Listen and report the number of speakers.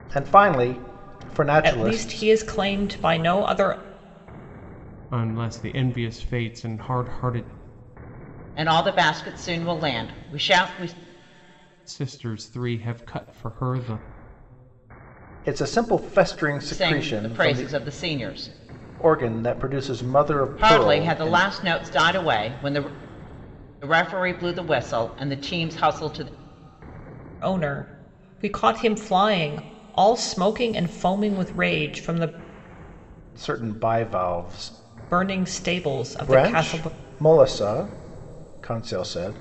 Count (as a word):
four